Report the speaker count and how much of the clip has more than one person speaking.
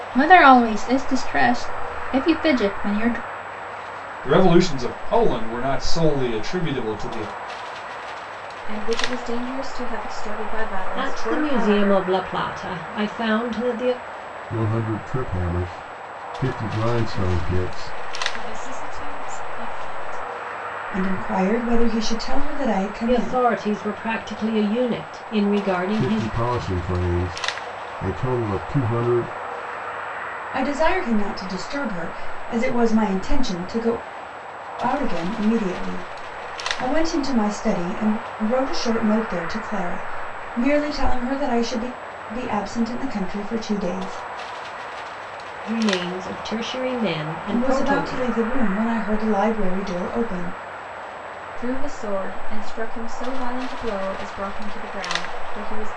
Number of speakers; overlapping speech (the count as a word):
seven, about 7%